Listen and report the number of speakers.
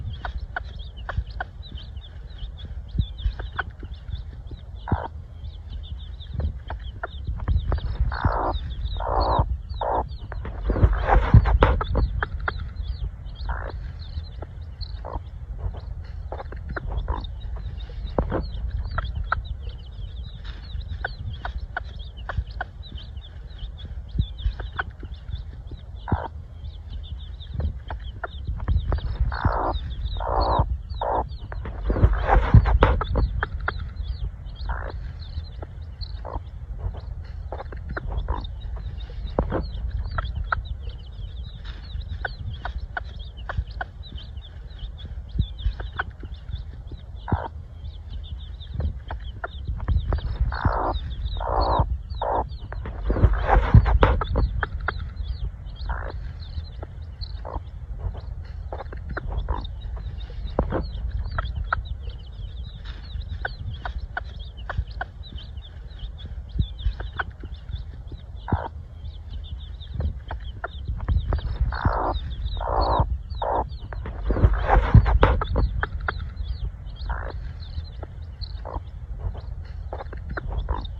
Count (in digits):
0